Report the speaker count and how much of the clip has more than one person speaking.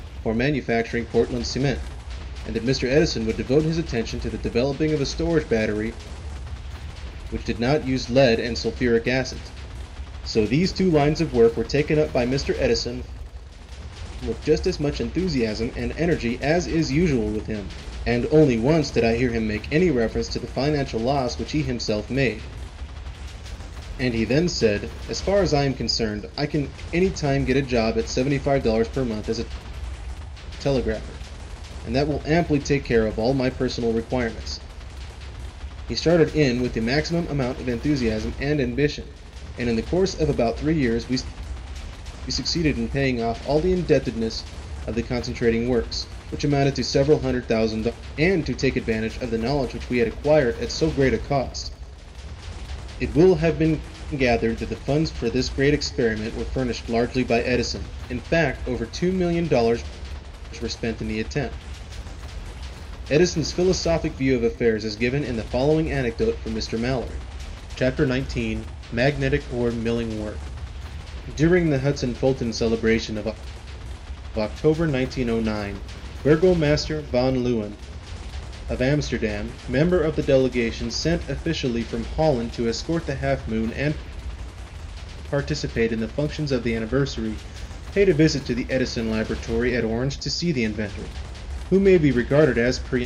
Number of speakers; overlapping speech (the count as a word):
one, no overlap